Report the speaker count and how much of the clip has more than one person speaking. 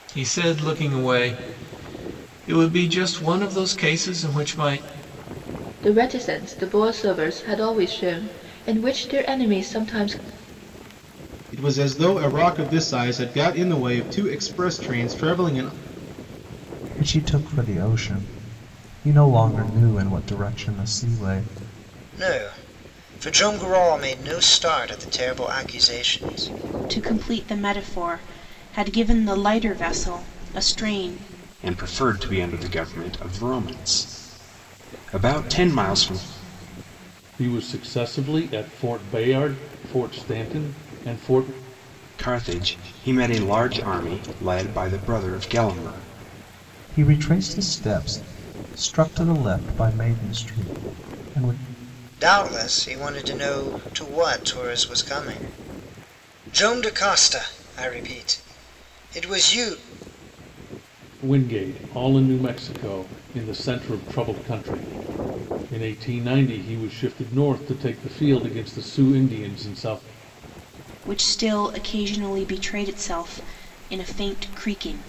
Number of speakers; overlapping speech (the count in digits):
8, no overlap